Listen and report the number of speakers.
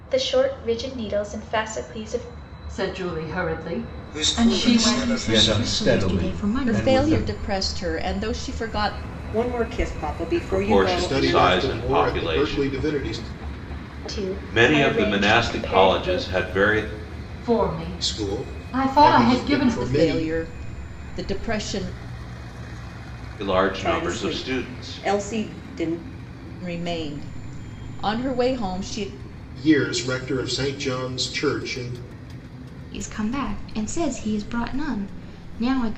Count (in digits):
9